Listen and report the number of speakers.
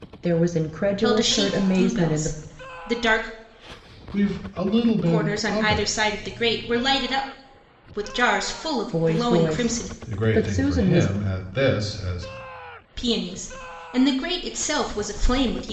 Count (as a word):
three